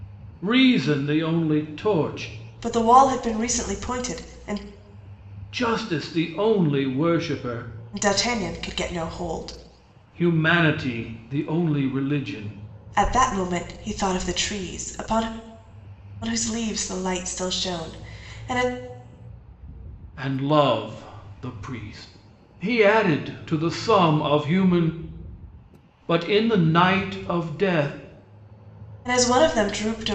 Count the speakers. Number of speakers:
two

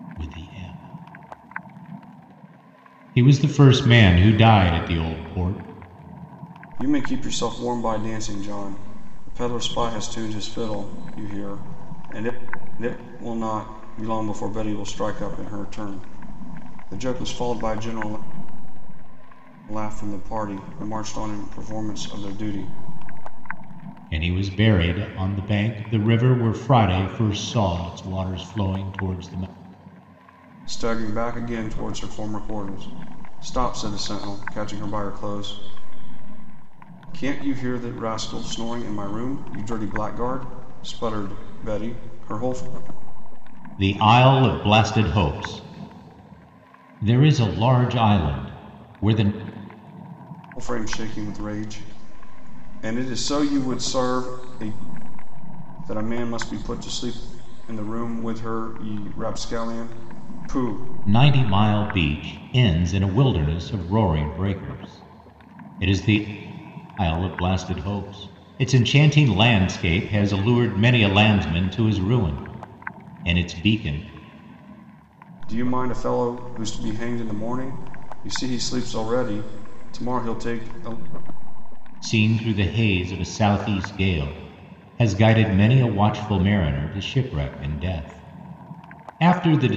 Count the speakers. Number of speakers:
two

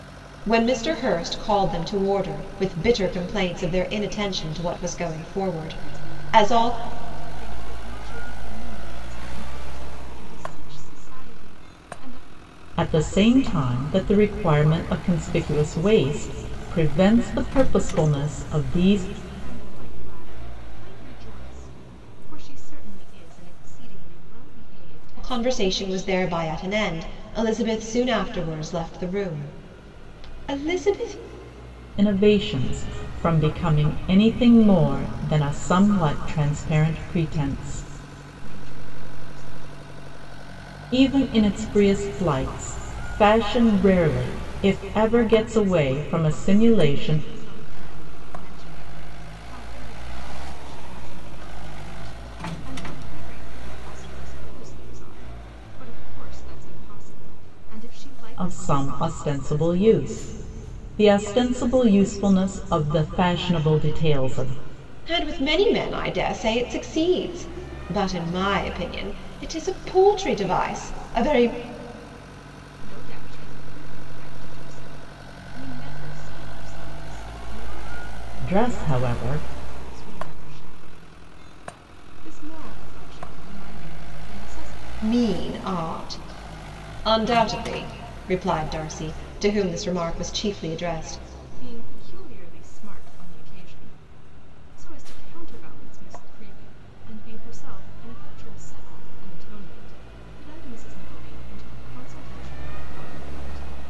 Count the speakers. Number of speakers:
three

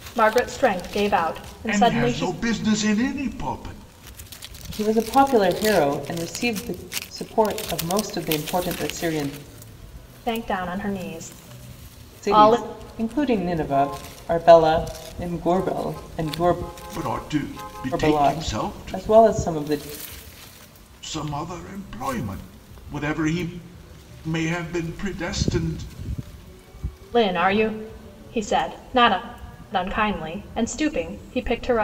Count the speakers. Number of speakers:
three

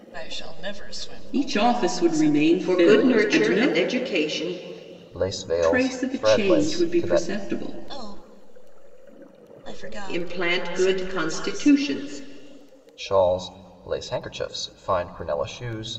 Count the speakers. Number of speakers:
four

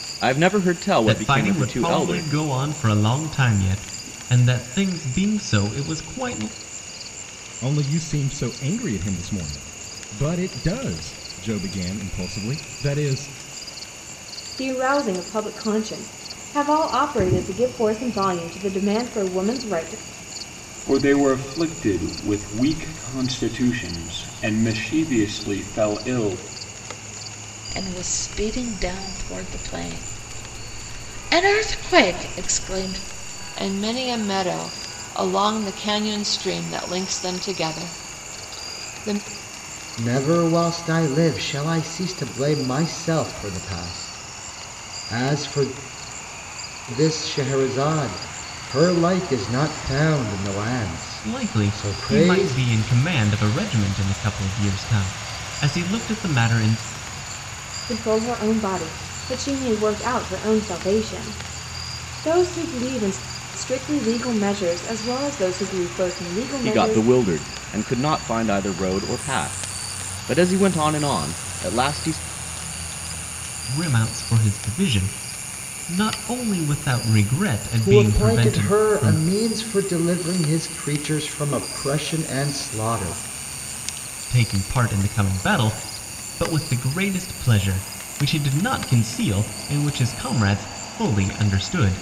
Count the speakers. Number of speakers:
eight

